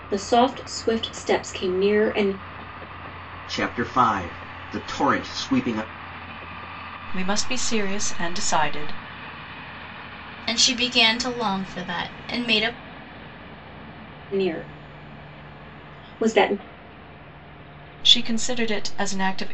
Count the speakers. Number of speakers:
4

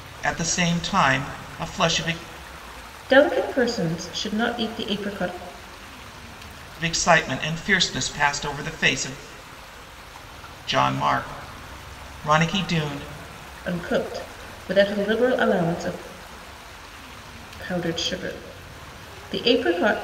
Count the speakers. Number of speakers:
2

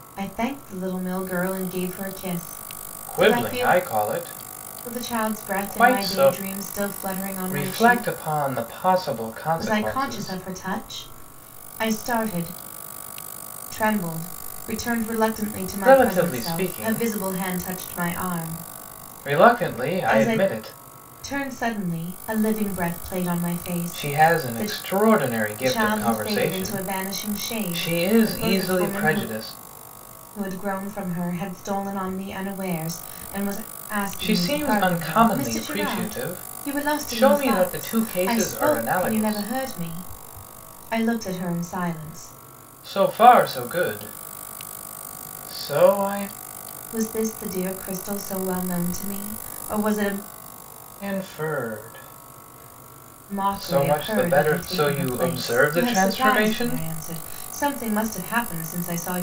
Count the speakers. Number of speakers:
2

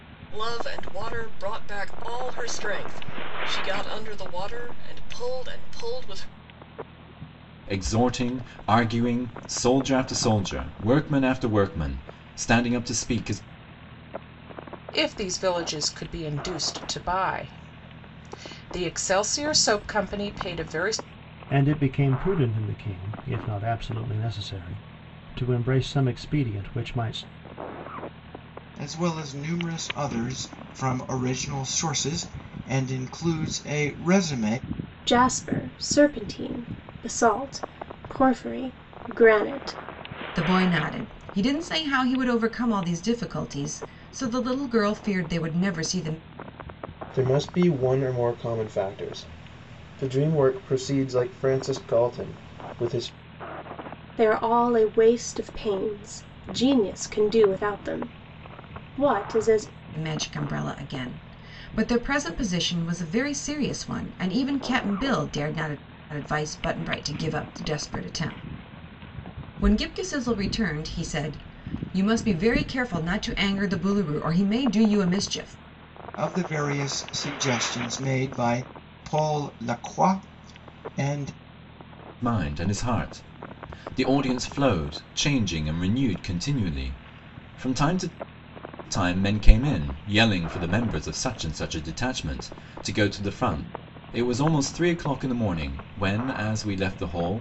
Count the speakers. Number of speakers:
8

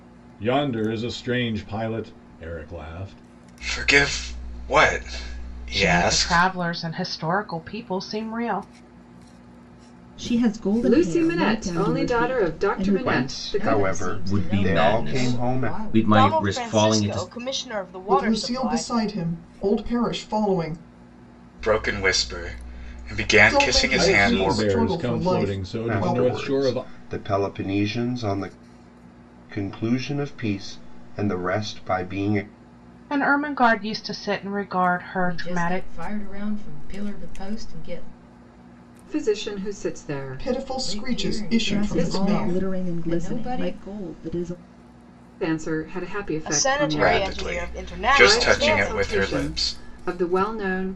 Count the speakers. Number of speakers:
10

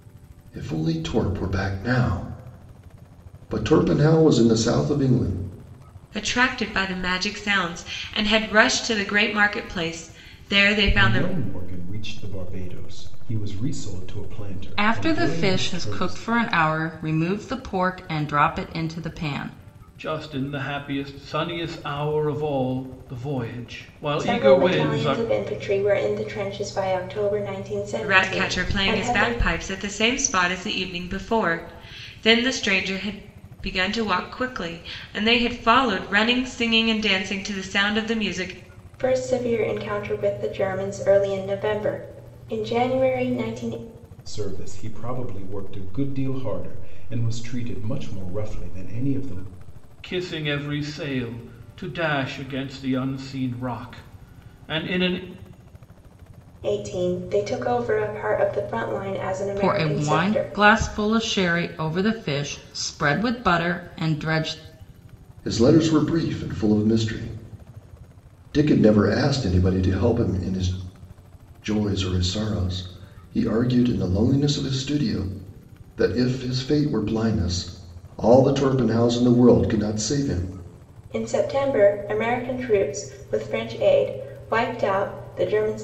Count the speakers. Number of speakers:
6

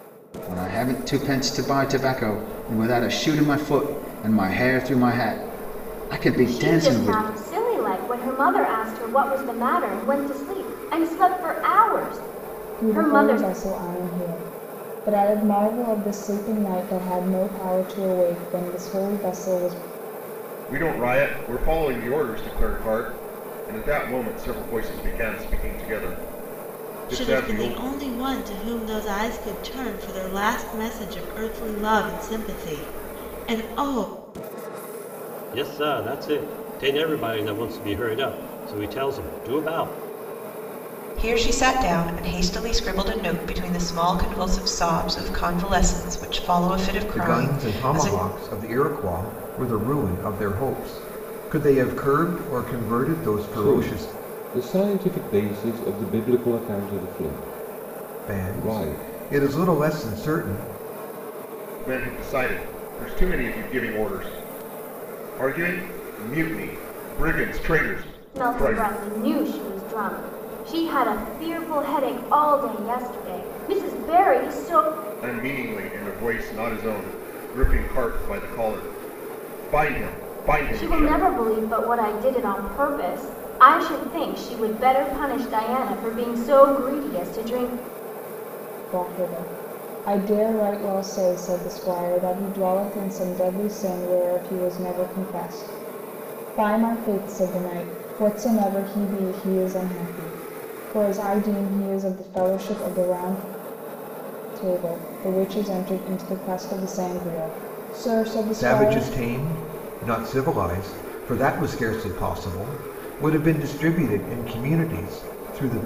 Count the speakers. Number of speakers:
9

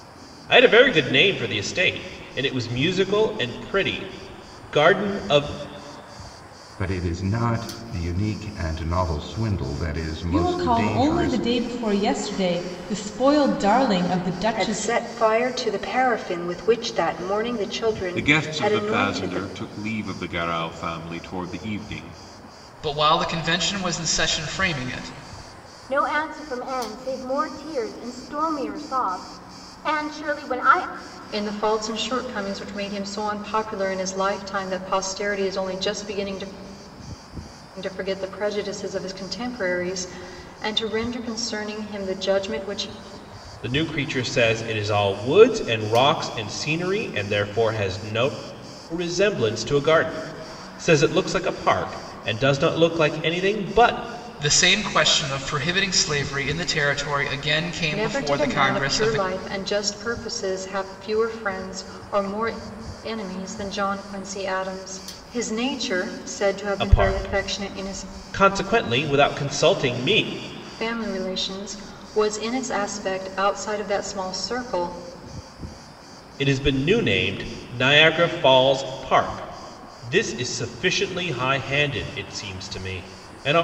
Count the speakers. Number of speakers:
8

